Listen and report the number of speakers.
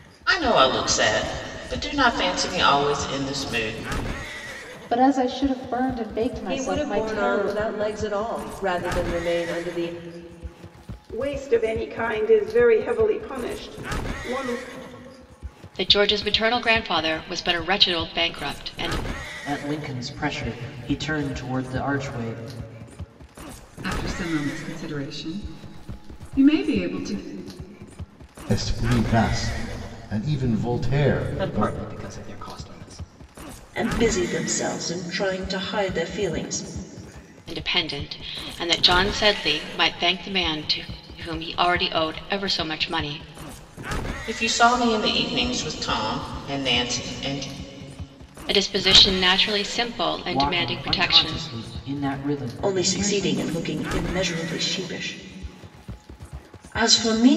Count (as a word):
ten